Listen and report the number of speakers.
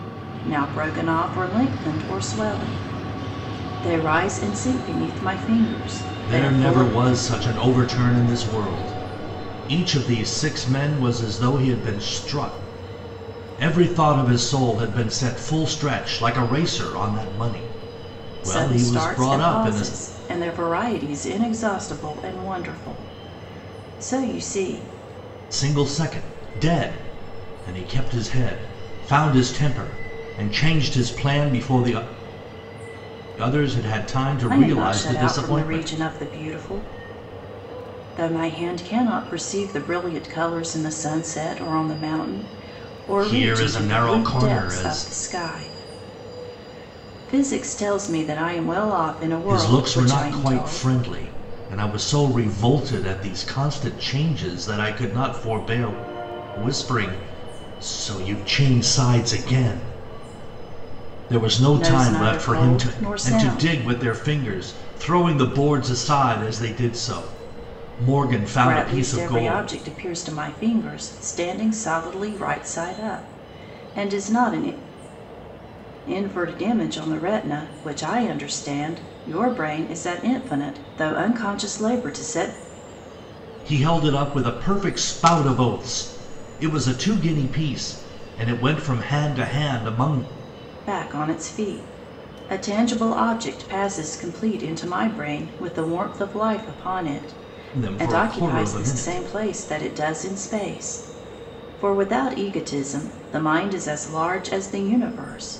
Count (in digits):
2